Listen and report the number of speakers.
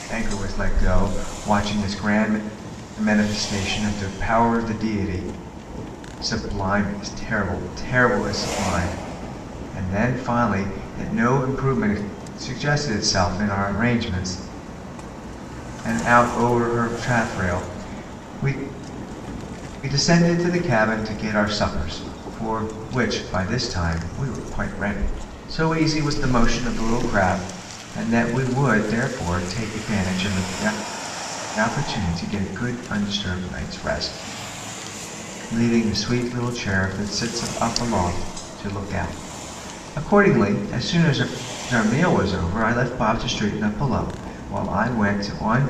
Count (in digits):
1